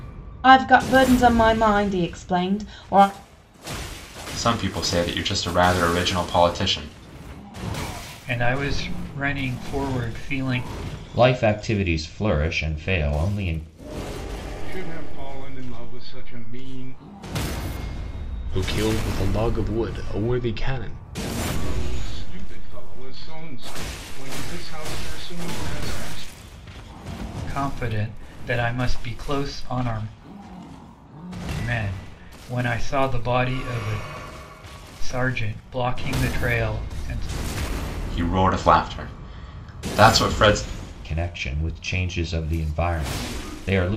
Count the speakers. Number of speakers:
6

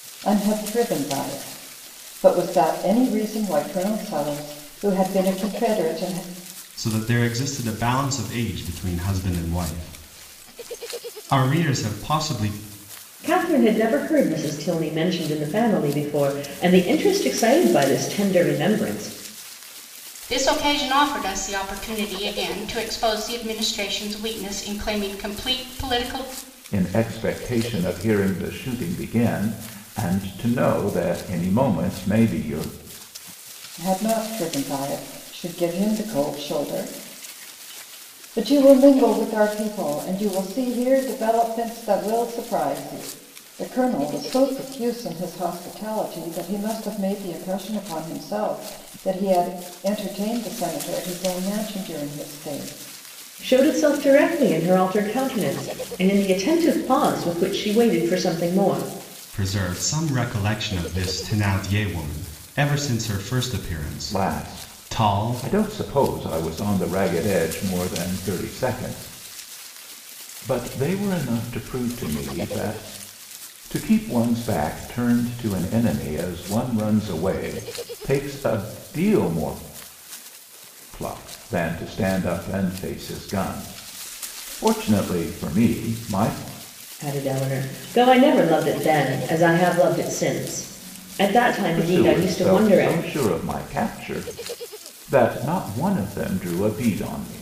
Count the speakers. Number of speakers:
5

